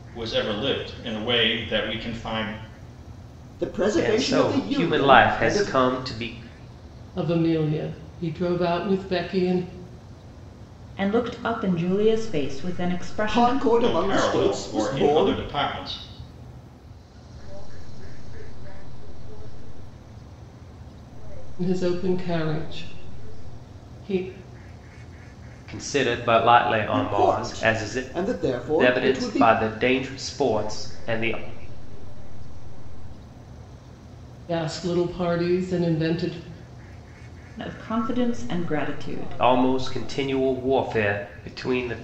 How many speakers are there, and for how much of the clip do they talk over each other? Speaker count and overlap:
six, about 29%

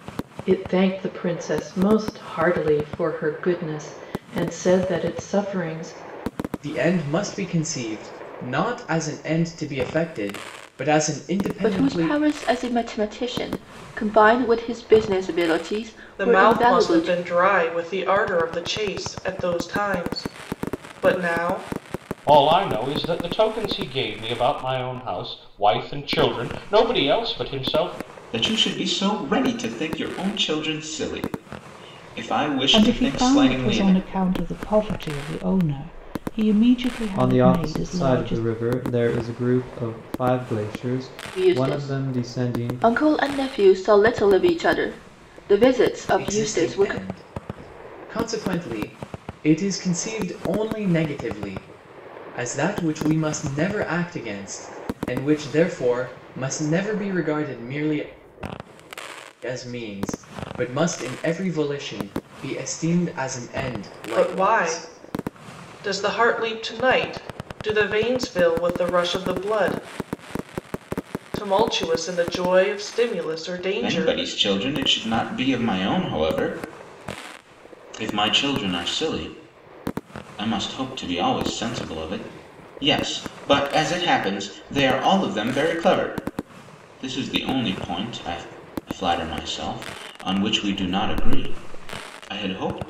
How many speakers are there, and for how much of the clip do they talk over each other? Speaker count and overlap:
eight, about 8%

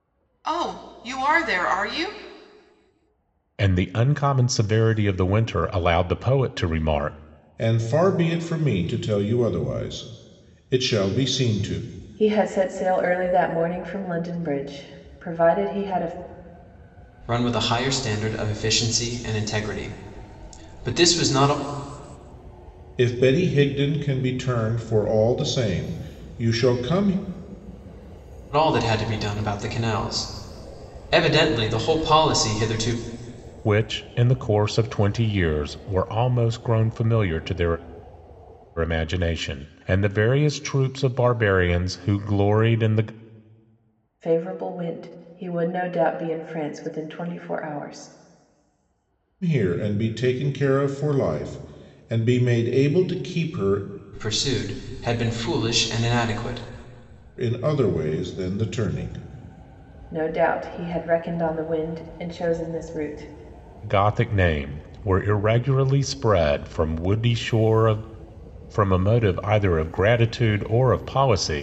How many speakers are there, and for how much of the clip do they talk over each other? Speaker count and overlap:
five, no overlap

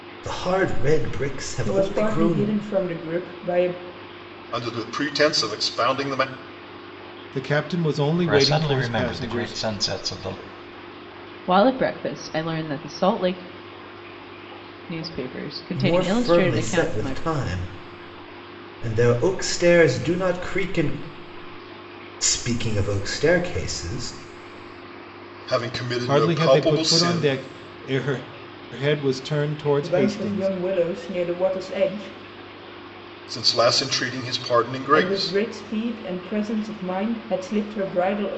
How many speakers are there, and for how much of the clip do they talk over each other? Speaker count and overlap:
six, about 17%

